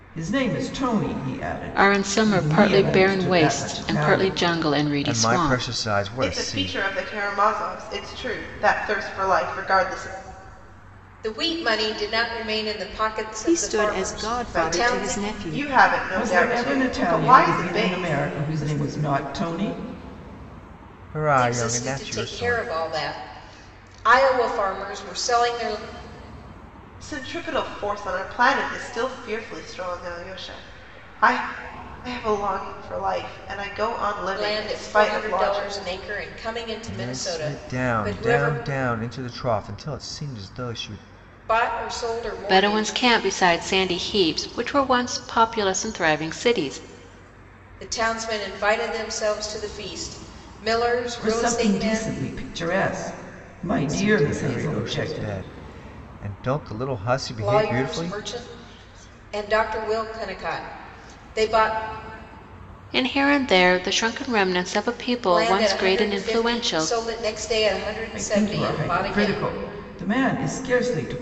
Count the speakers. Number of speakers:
six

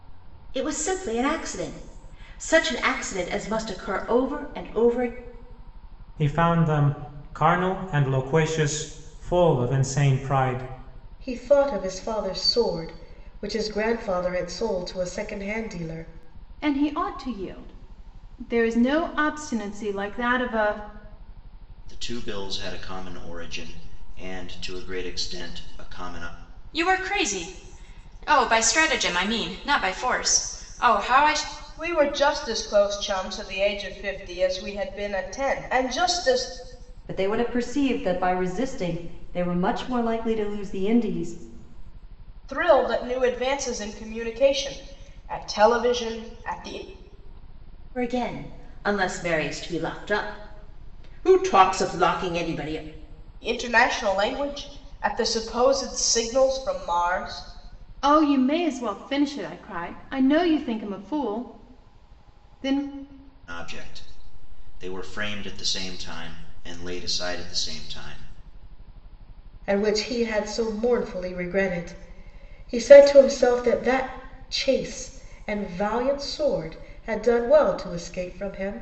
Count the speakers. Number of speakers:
eight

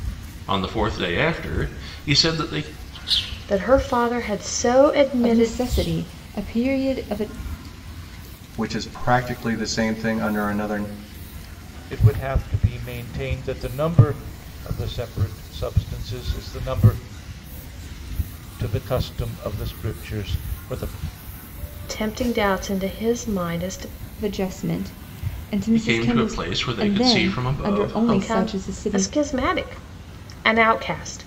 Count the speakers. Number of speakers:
five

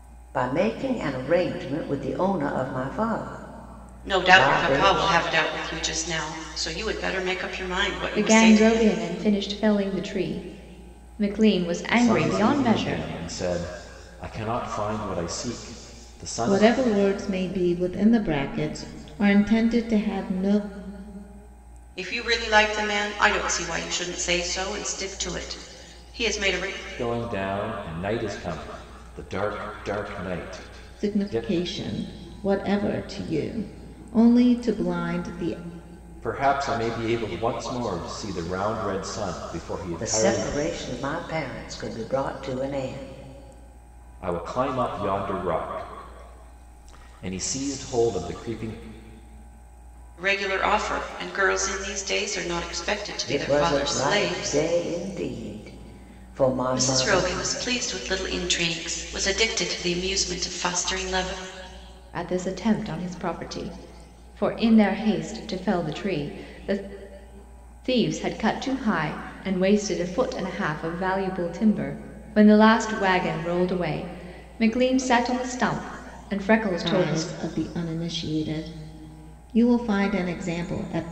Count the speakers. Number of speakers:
five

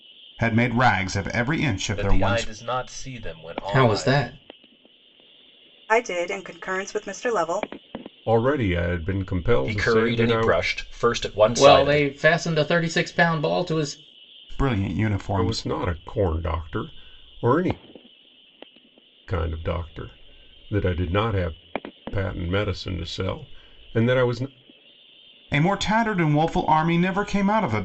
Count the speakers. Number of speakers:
six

